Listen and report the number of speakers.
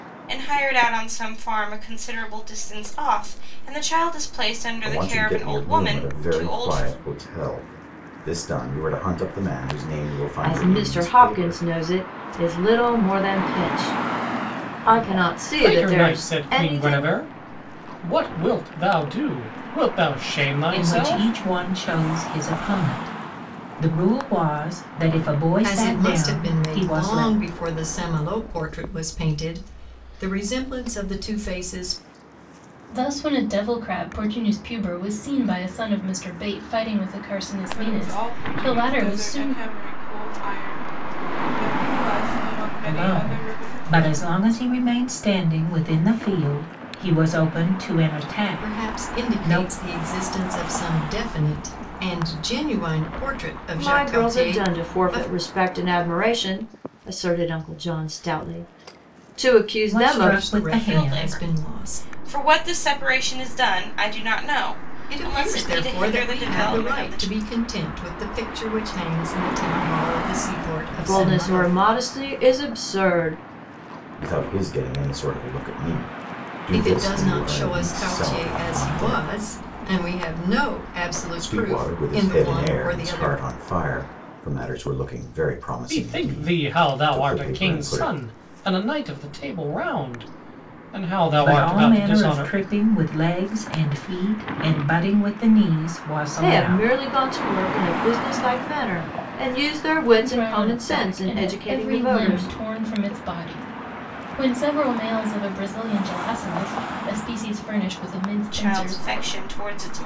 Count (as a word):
eight